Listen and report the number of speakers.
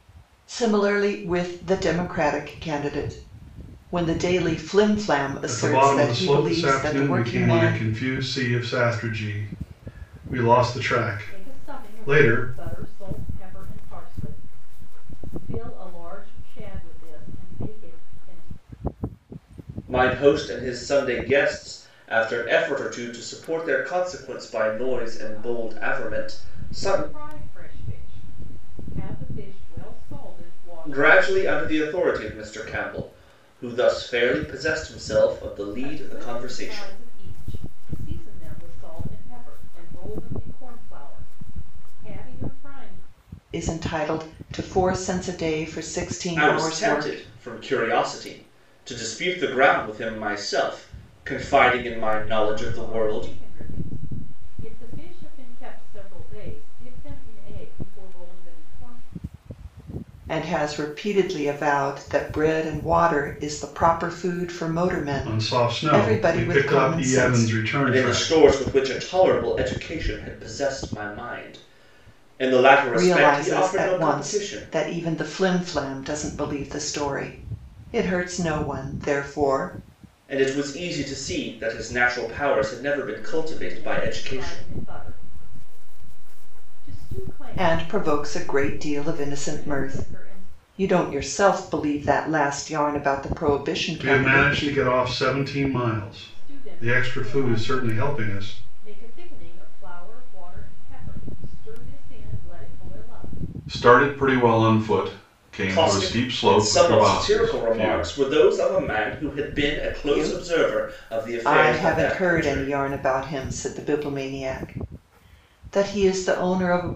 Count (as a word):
four